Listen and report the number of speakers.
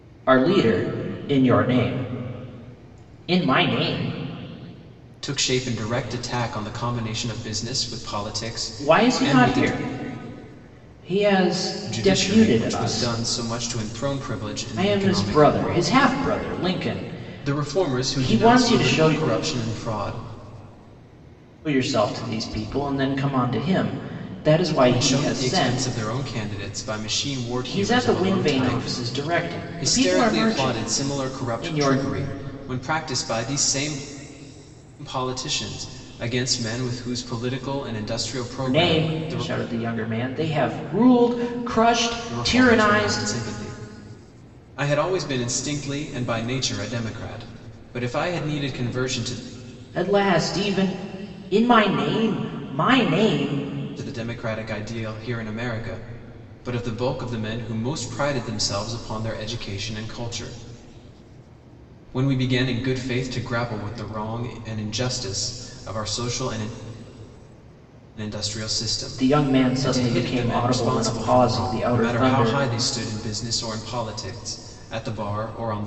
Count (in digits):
2